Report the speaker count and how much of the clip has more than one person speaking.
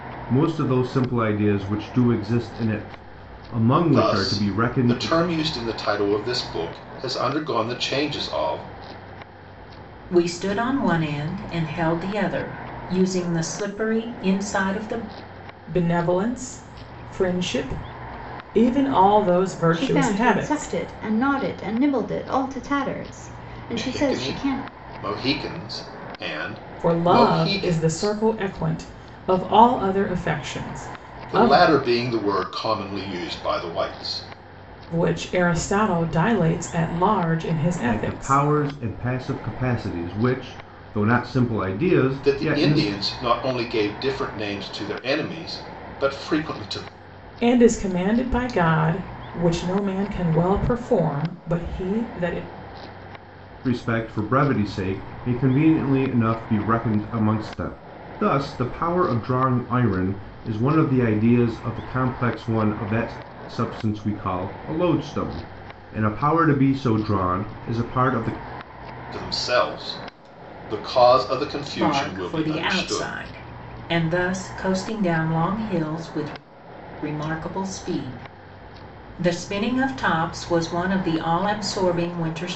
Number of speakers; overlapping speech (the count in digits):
5, about 10%